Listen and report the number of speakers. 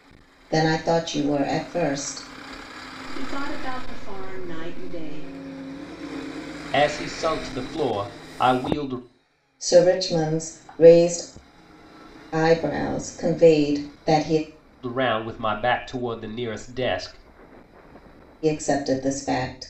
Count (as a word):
three